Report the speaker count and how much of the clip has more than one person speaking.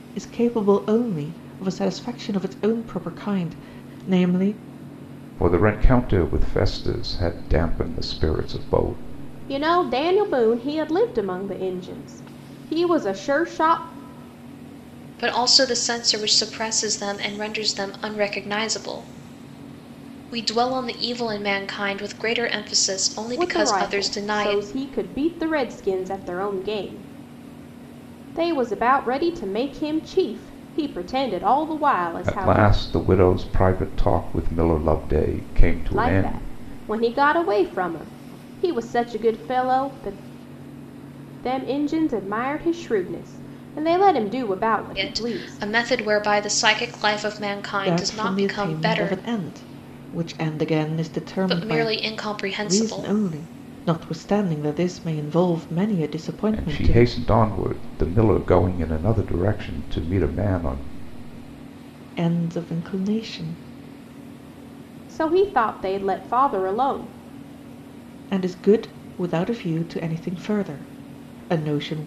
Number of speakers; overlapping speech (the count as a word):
four, about 9%